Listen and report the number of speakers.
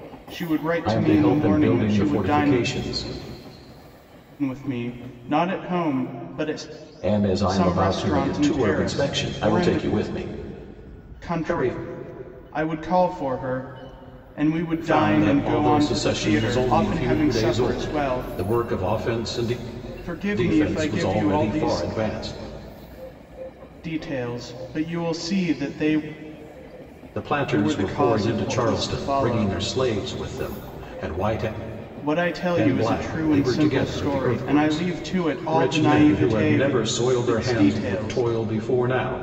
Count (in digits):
2